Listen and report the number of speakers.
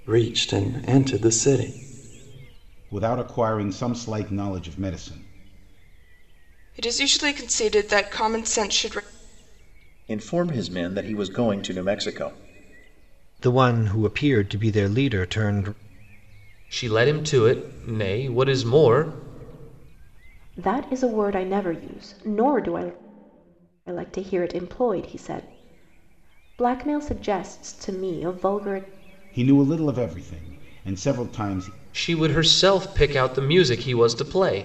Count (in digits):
7